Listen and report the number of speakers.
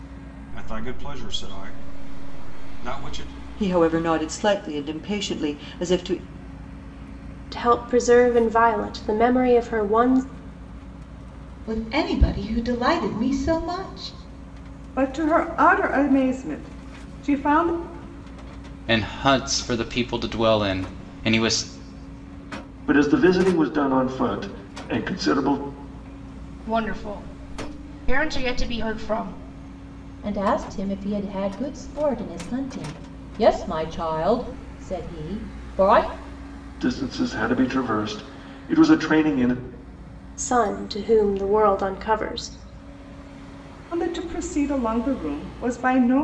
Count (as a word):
nine